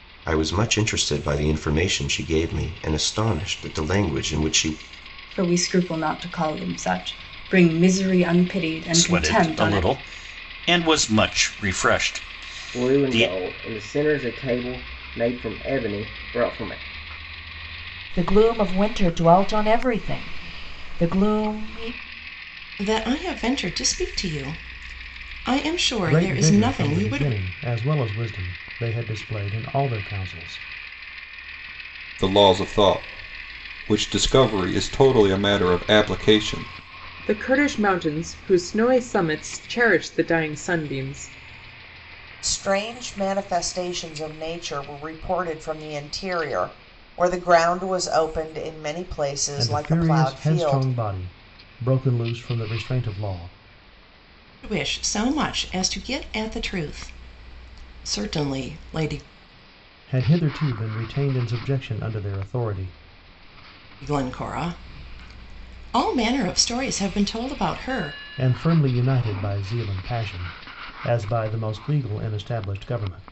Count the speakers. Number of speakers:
10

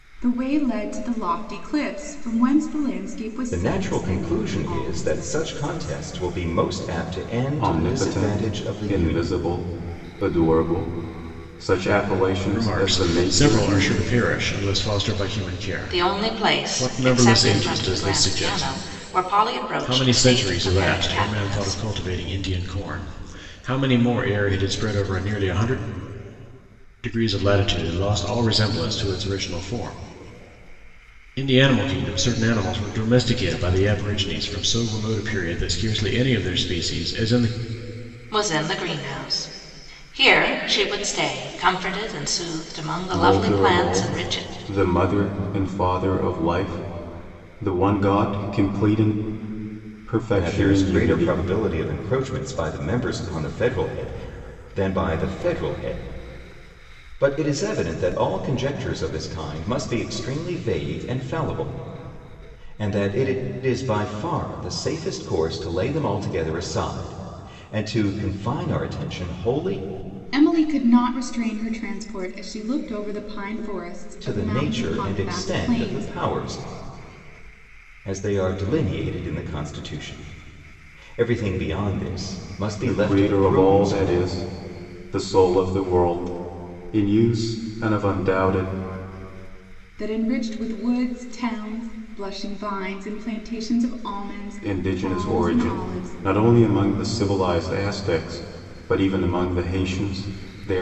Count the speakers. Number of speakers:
5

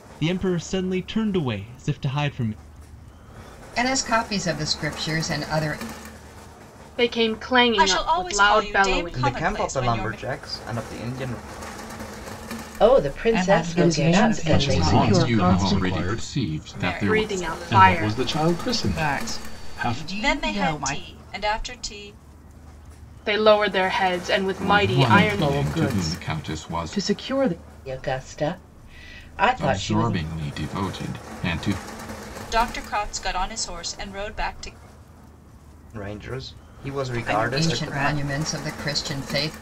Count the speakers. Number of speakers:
10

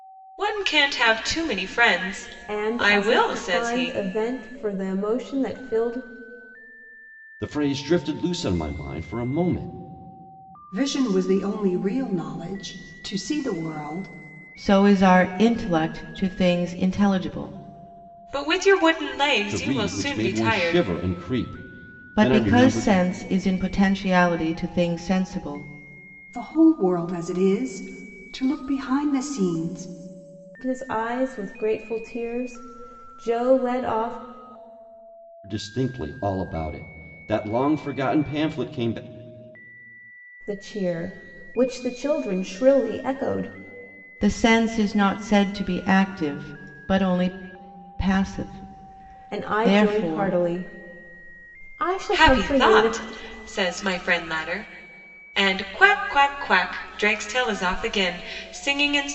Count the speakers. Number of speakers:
5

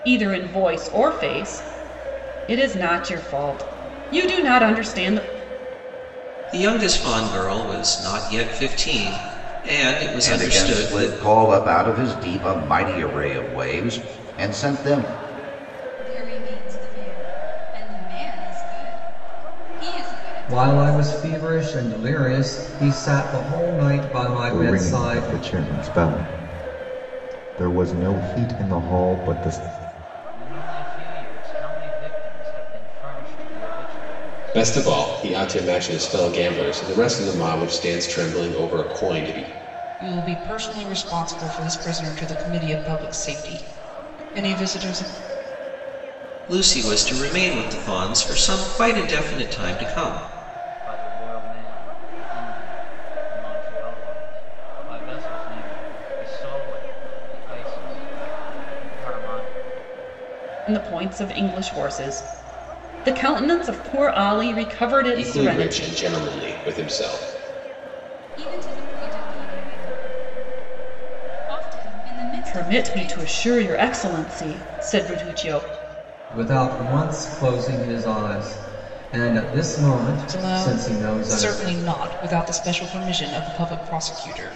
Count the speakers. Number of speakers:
9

